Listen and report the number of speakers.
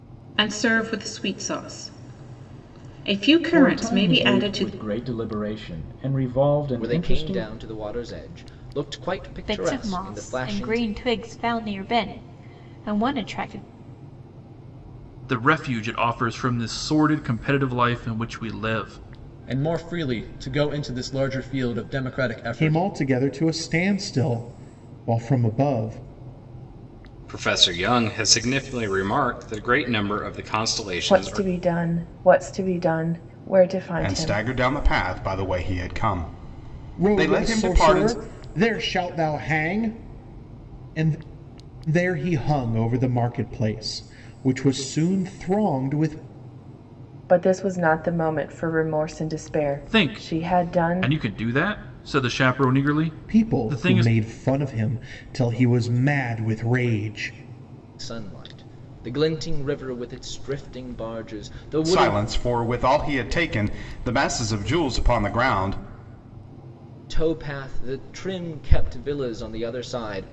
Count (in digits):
10